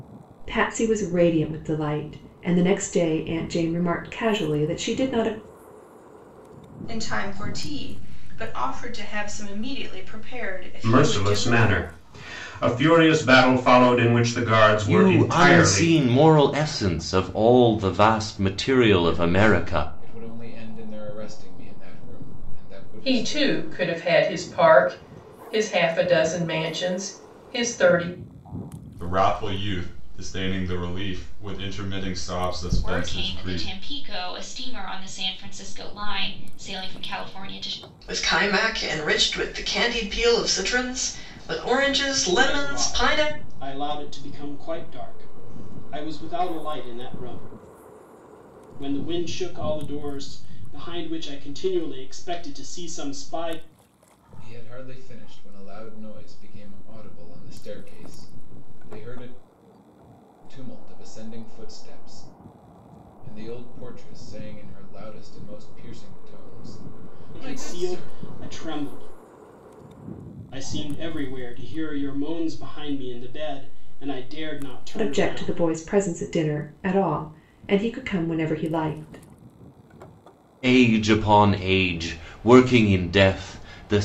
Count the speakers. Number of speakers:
ten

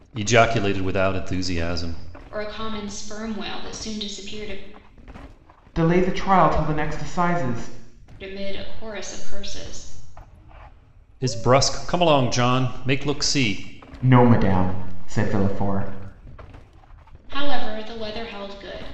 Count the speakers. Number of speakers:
three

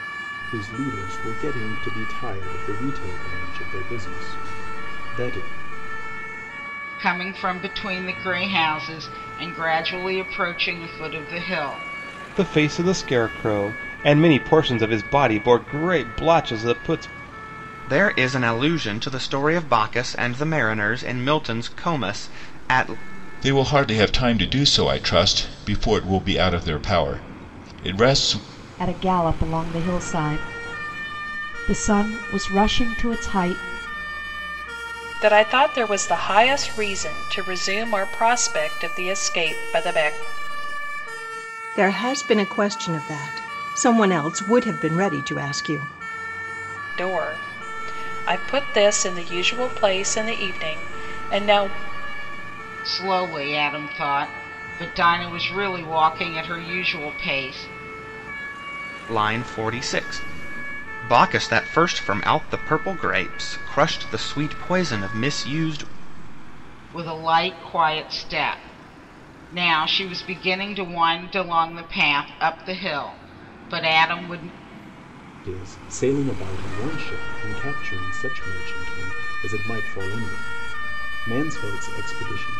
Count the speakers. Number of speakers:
eight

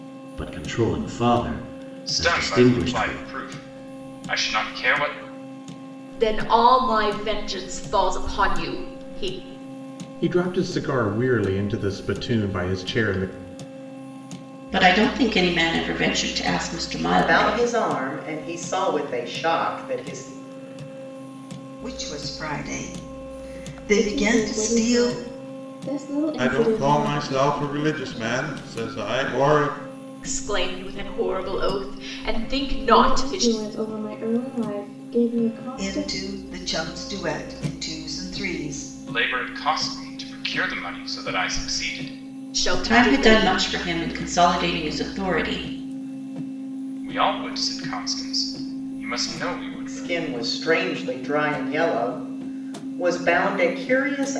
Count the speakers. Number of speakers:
nine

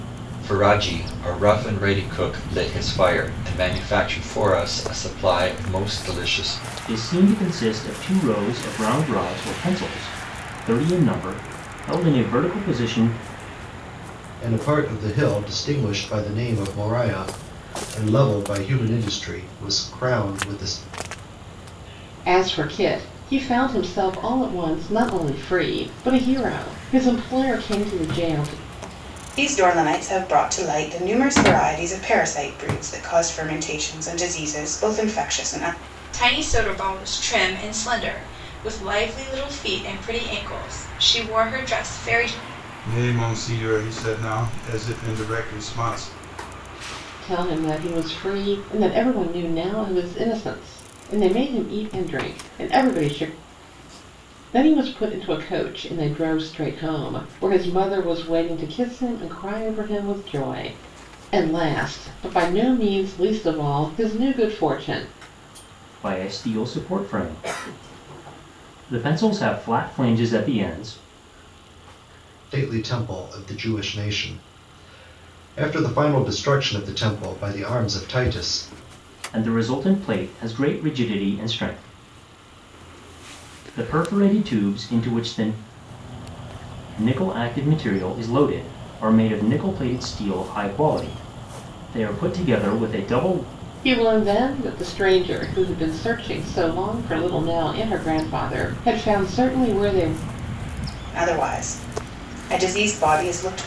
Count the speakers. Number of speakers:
seven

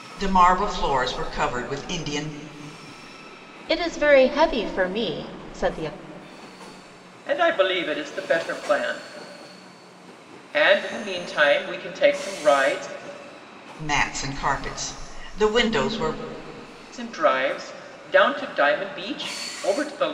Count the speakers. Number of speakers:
three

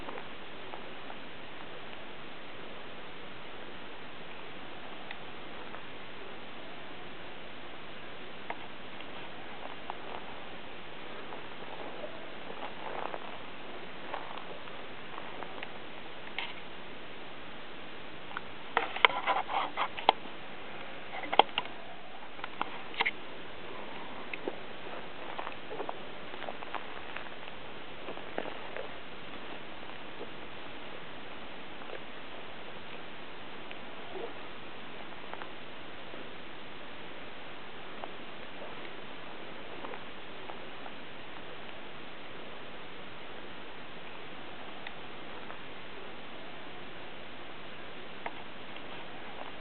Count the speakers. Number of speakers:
zero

